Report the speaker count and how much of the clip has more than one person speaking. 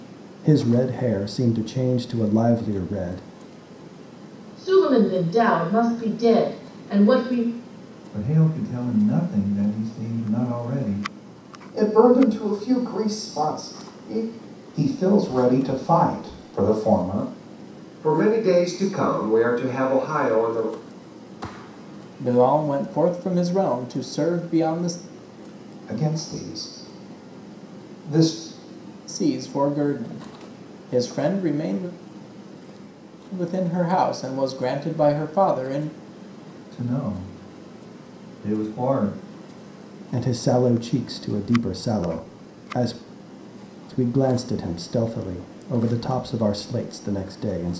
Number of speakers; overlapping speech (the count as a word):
seven, no overlap